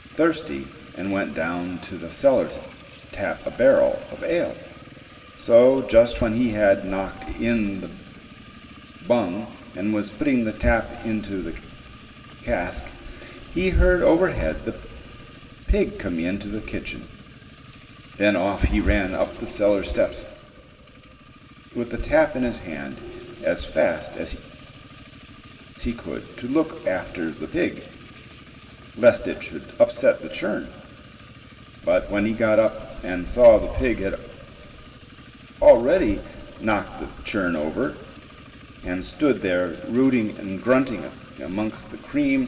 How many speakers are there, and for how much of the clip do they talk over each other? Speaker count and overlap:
one, no overlap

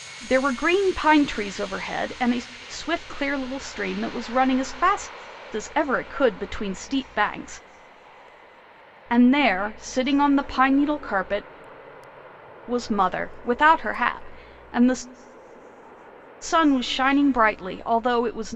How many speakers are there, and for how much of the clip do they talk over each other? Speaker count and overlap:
one, no overlap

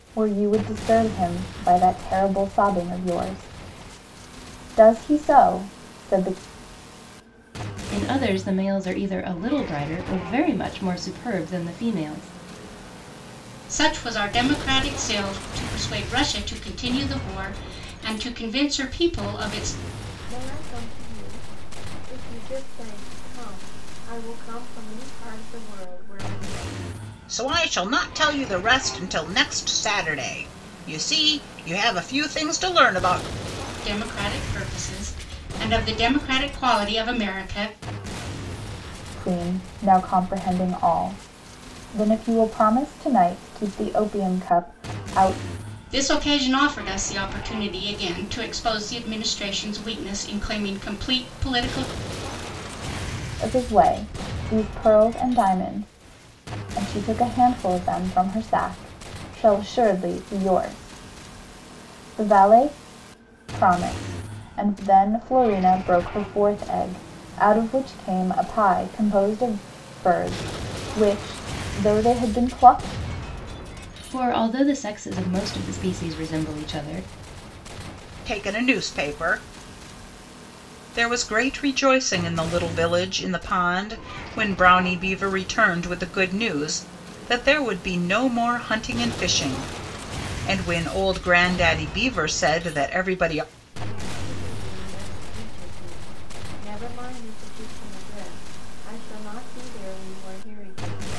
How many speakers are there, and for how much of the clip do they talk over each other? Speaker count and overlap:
five, no overlap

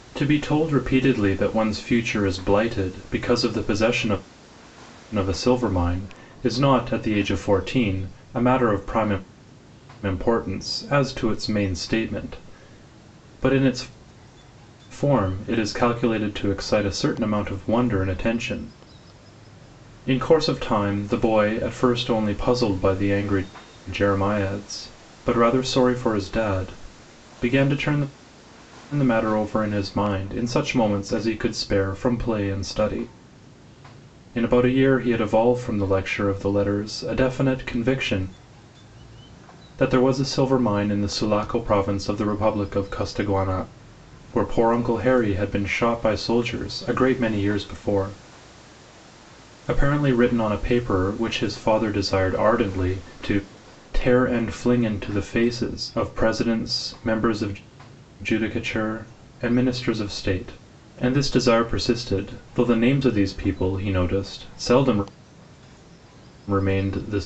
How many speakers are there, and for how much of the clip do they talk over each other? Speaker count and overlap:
one, no overlap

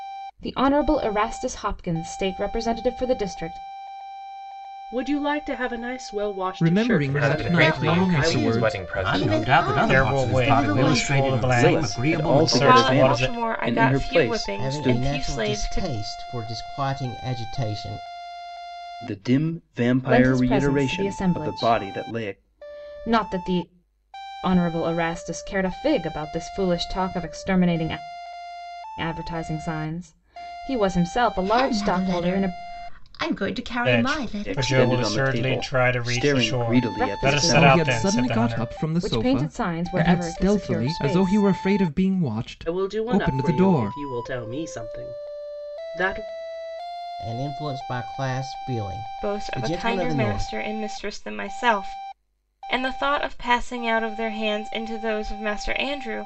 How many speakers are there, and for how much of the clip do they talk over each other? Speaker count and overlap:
ten, about 41%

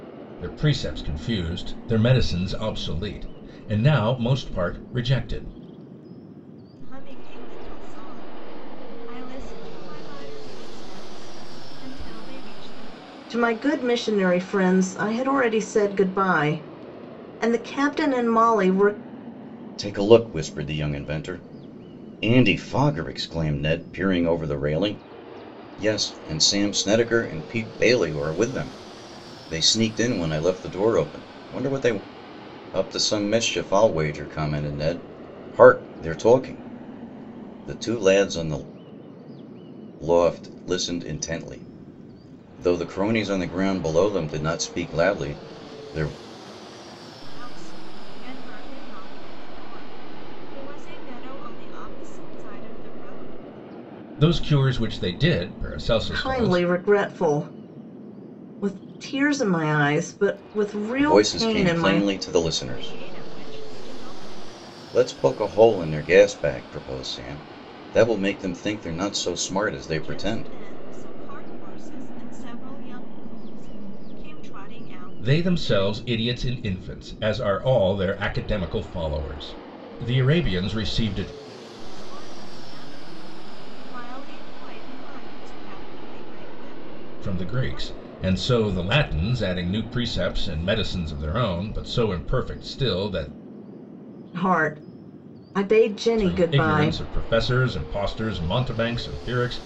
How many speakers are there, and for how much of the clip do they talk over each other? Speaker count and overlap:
four, about 5%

